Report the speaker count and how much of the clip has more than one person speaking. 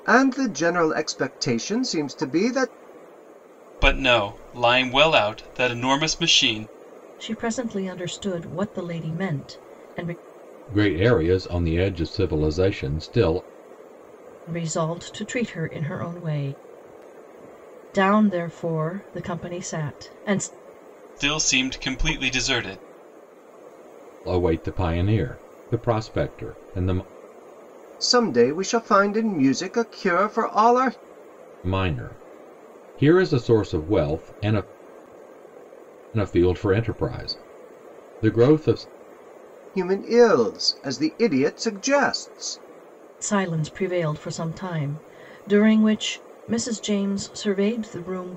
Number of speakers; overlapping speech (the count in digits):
4, no overlap